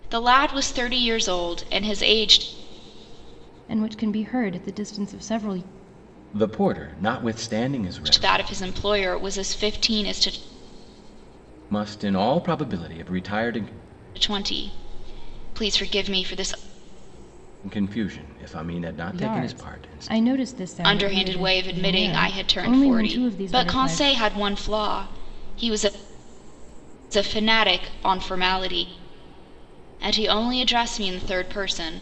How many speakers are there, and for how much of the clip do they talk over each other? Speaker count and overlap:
three, about 13%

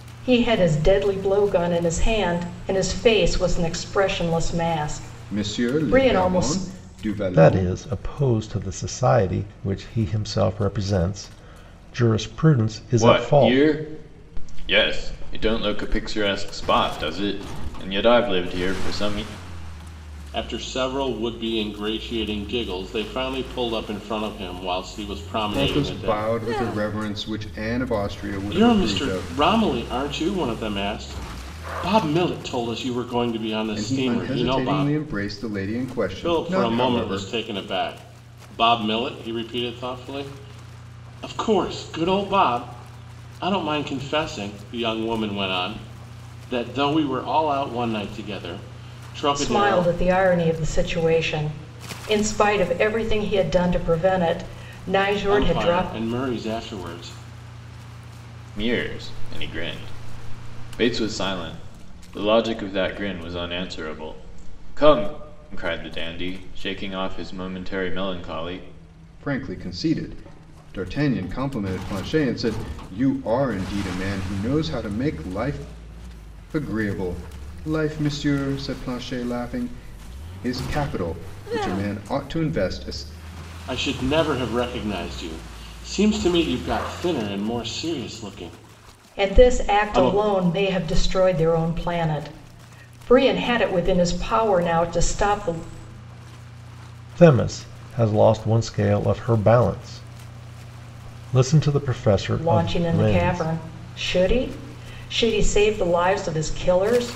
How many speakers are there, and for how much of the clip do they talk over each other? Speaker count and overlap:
five, about 9%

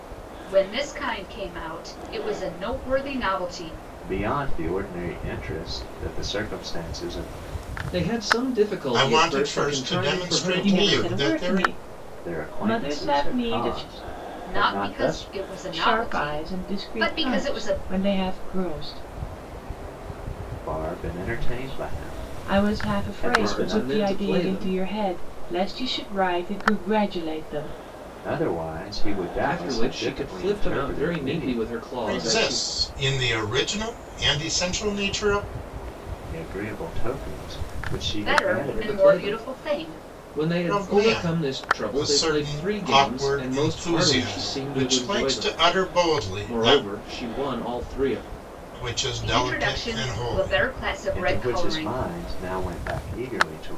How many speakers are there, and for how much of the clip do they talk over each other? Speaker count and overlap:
five, about 45%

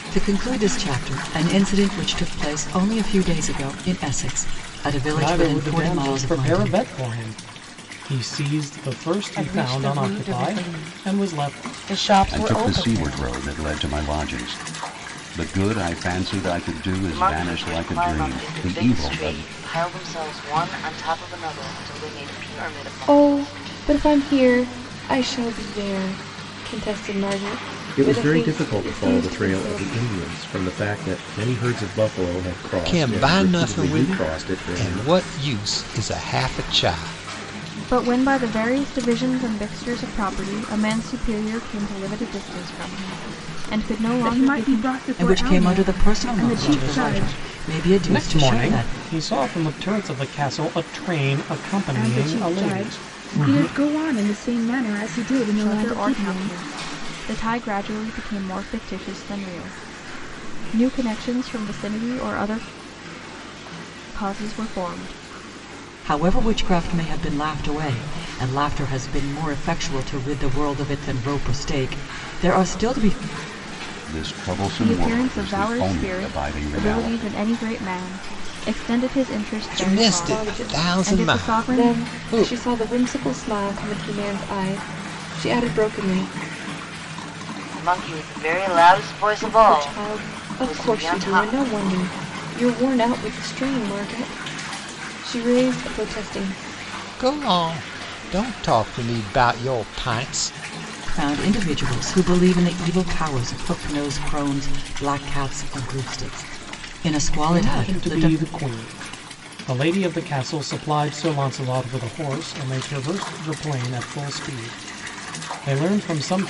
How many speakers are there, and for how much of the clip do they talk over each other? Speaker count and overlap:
ten, about 24%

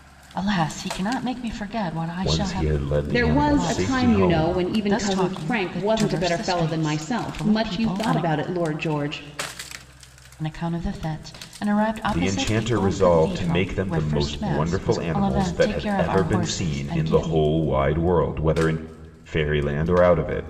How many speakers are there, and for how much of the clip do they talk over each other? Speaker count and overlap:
three, about 54%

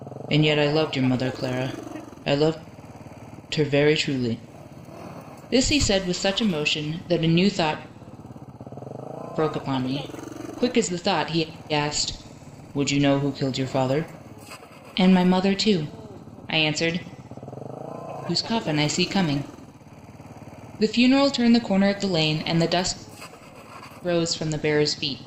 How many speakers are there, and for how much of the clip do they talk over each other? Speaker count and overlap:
one, no overlap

